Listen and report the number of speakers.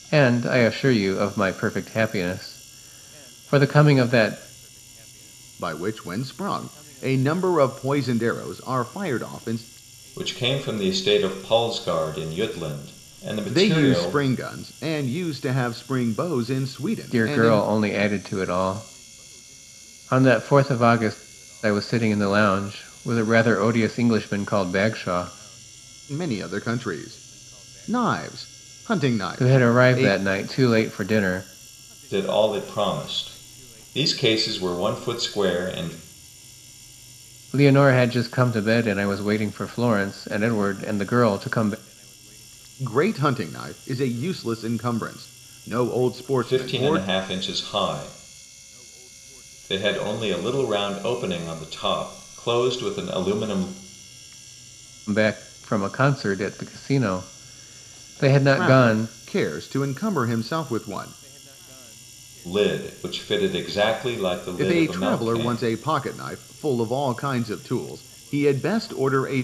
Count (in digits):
3